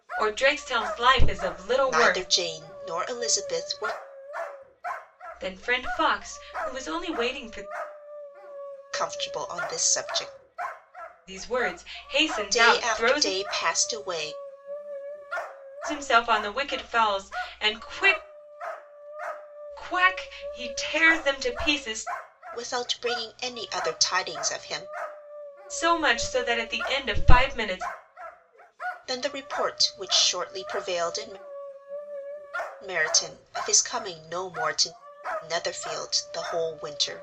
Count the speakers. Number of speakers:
two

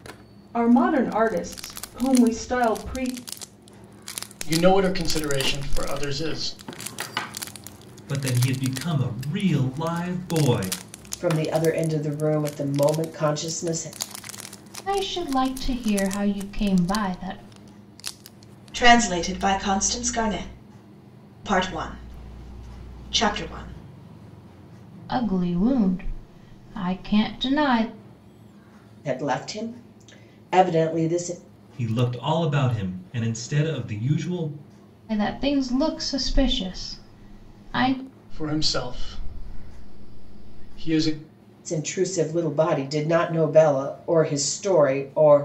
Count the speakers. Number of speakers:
six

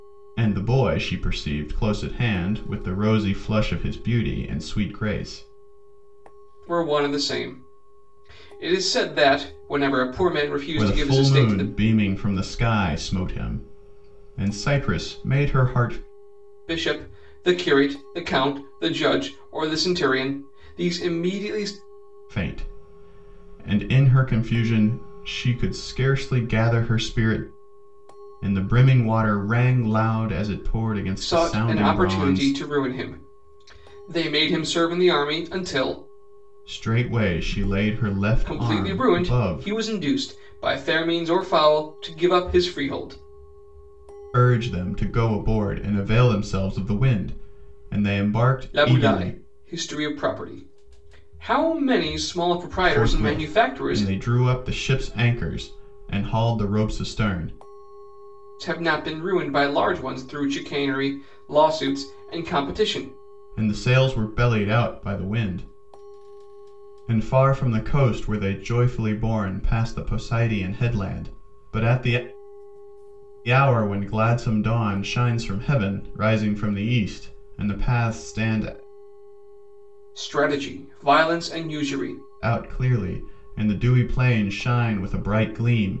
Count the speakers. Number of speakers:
two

